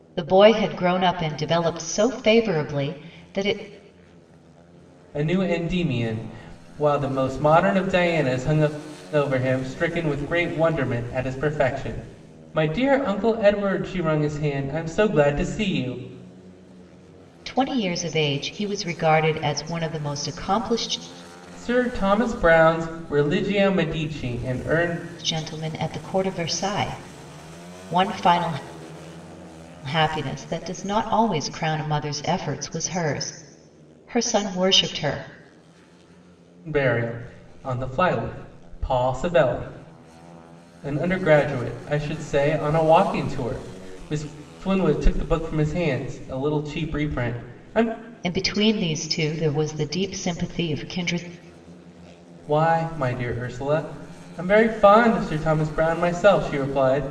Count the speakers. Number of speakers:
two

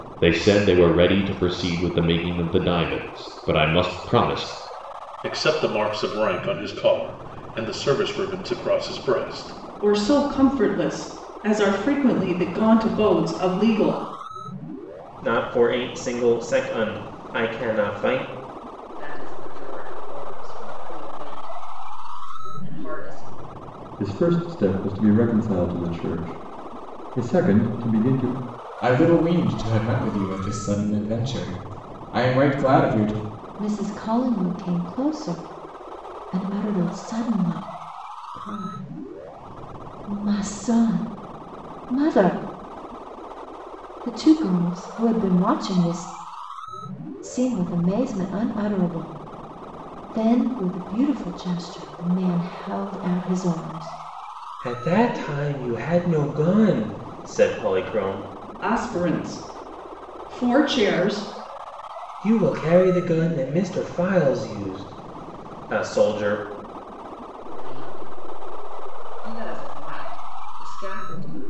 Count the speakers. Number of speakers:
eight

